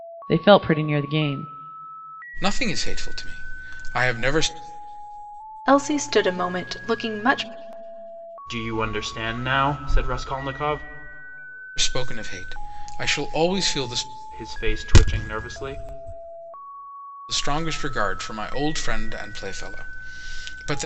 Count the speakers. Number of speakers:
4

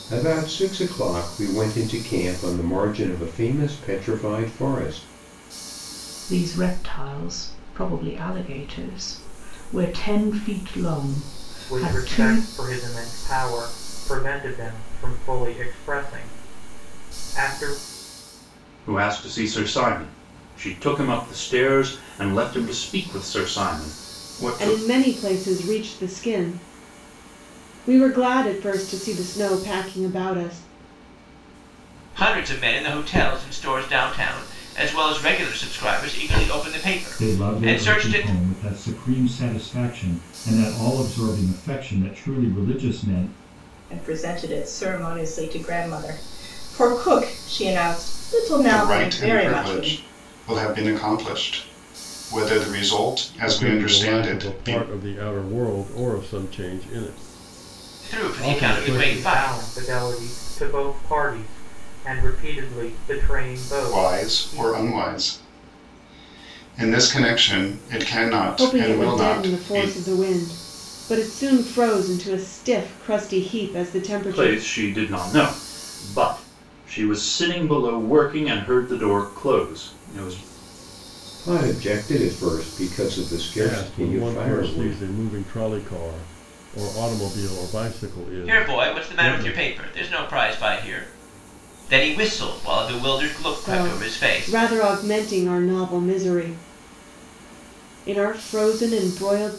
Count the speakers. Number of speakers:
10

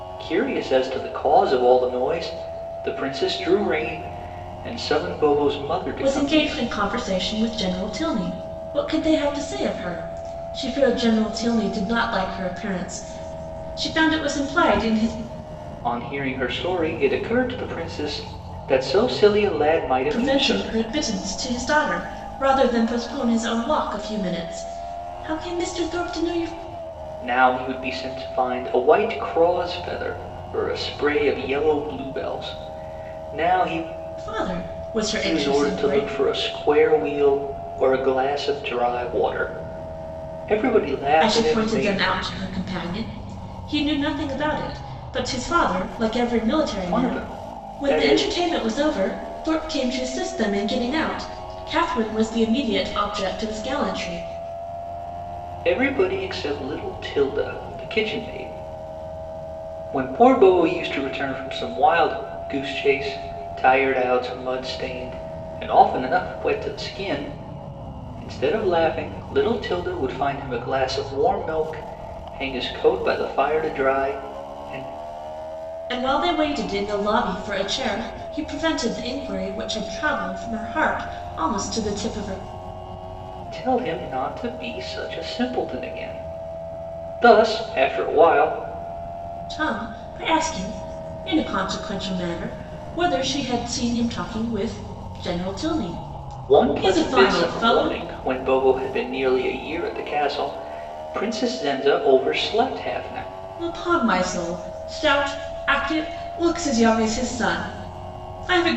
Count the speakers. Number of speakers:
2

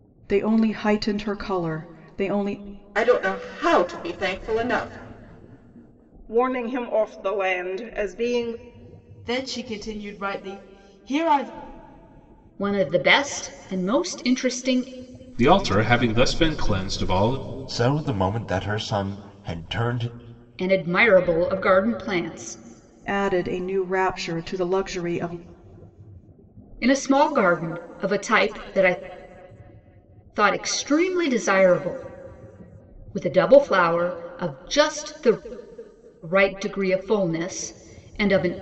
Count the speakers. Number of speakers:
7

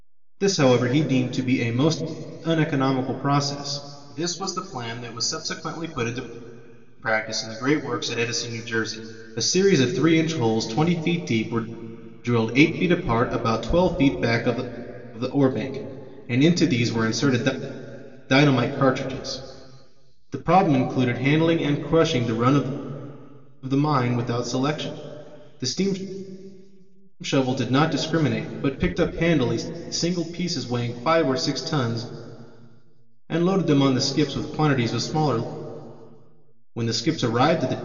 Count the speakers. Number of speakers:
1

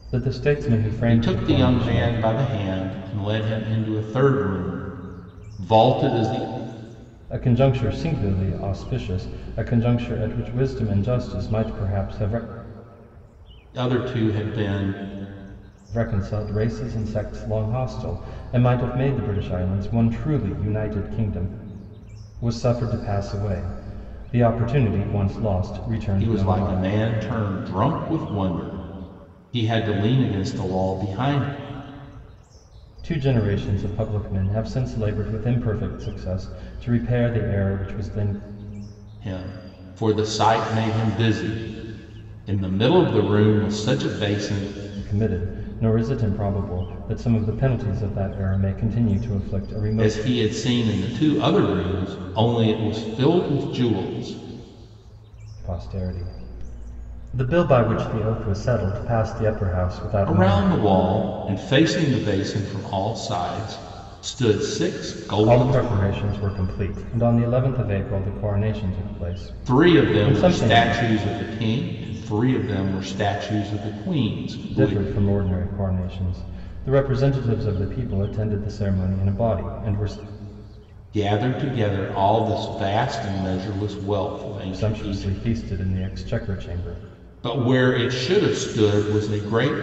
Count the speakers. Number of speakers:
2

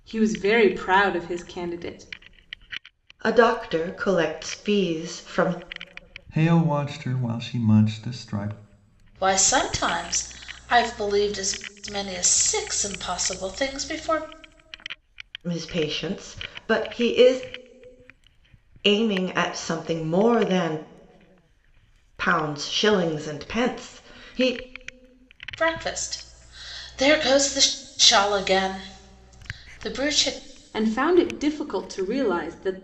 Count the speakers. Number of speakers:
4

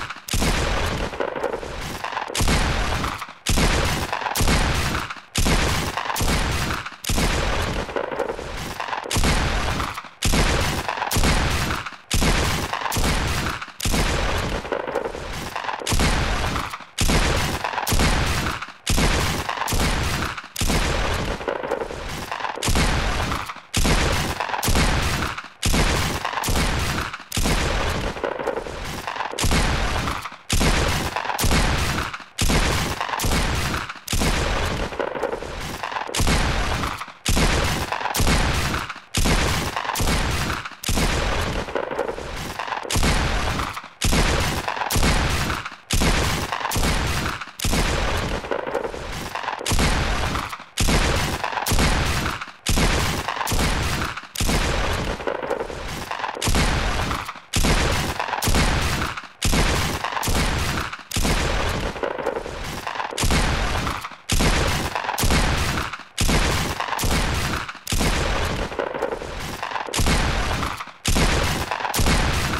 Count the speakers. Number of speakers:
0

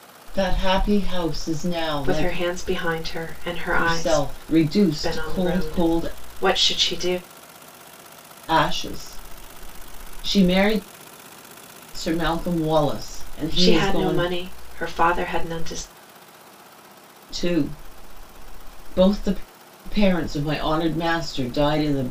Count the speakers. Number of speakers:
2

